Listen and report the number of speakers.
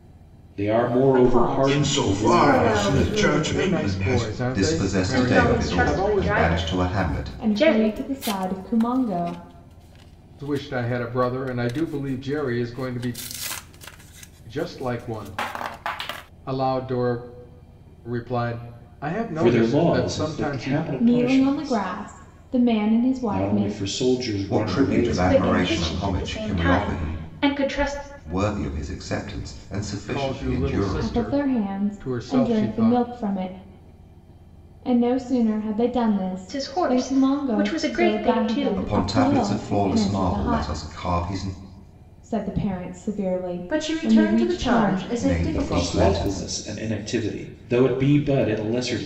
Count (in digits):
7